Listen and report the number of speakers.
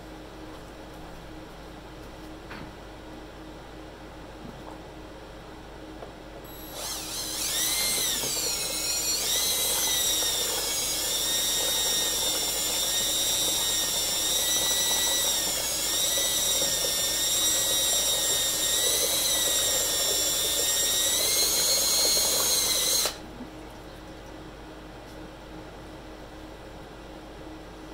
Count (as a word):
zero